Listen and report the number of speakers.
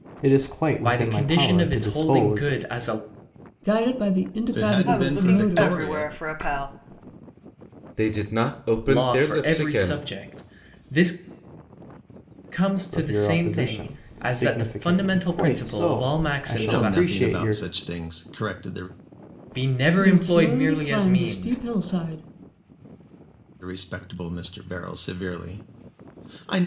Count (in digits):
6